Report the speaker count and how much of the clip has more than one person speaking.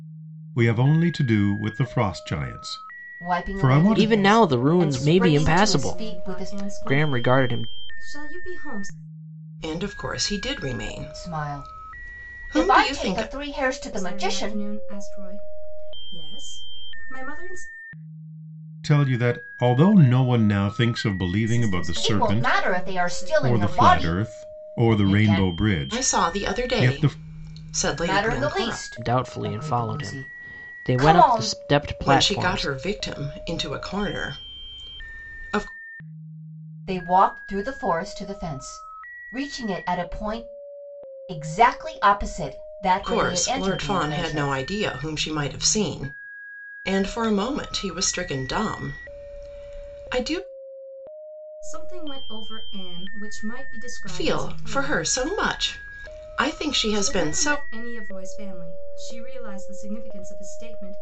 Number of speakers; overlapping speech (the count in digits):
5, about 33%